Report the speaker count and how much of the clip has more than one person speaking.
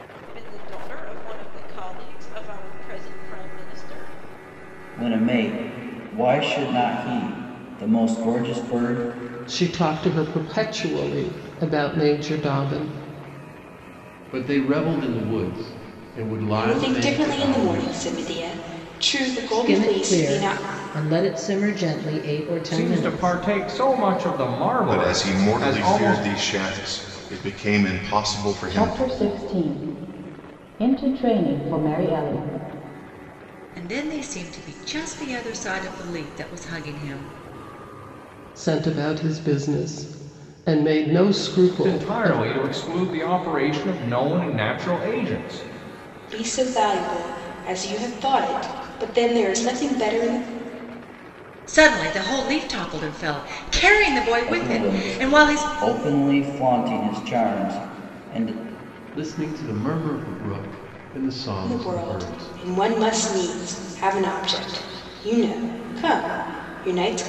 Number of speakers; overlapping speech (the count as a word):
ten, about 12%